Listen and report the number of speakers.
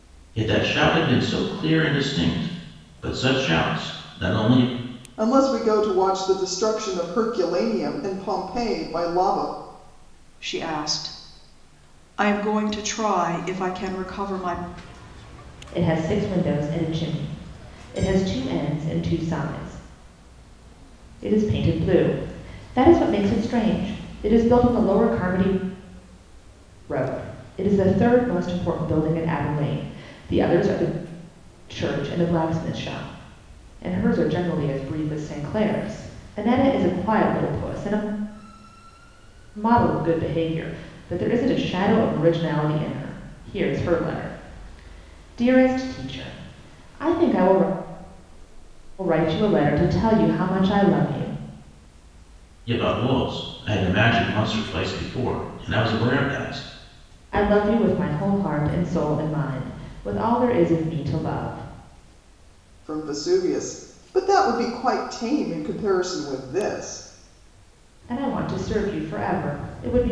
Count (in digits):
4